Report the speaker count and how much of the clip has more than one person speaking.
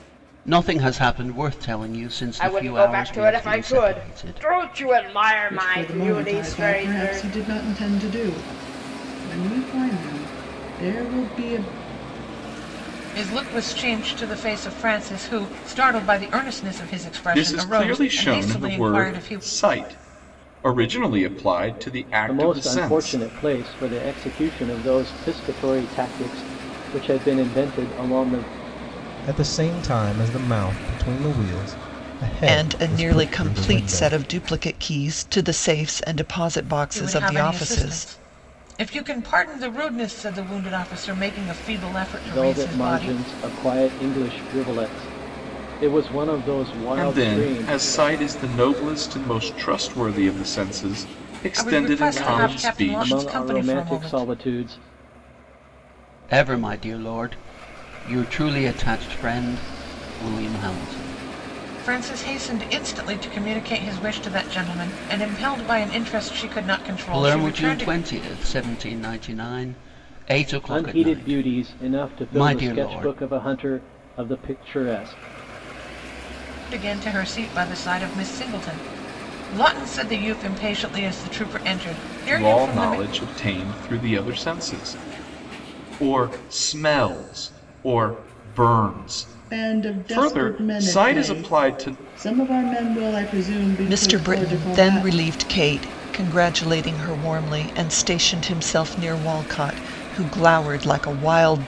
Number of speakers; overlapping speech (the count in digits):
8, about 23%